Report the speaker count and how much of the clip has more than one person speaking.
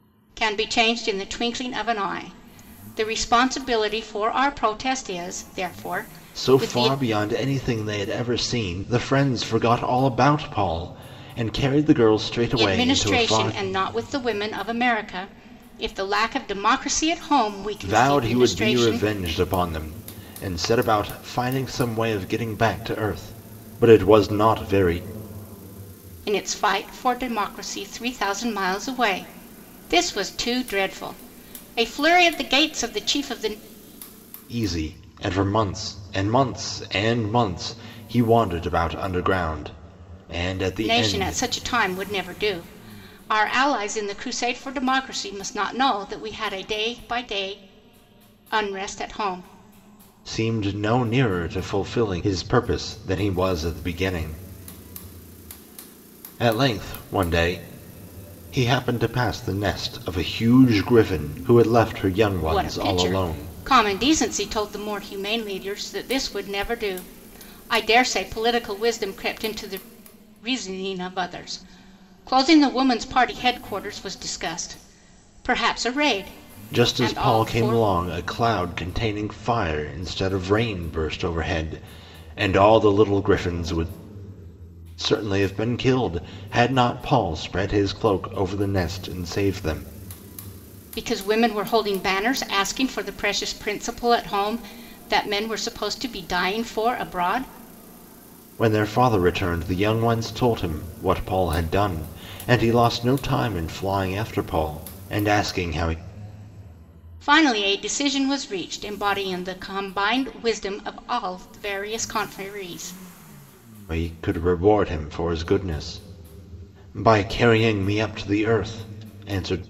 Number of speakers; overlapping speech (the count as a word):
two, about 5%